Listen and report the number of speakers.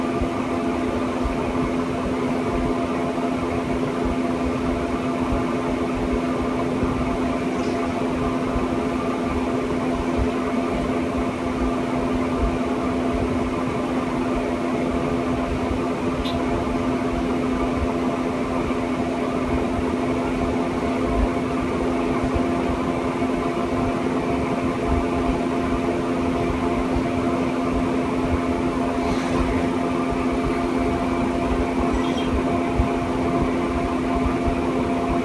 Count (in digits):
0